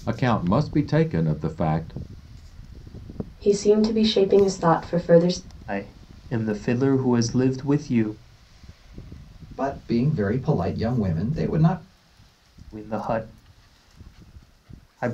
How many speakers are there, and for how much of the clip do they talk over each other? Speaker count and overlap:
four, no overlap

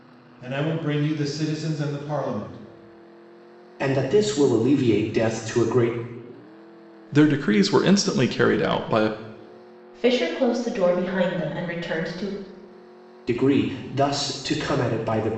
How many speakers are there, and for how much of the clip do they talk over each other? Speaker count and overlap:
four, no overlap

